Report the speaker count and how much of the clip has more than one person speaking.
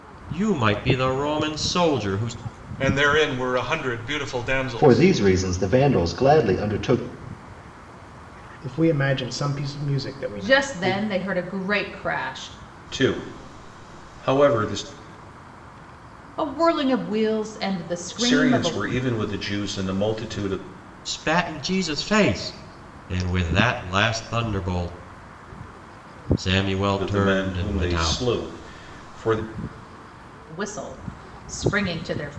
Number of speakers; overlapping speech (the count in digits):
6, about 9%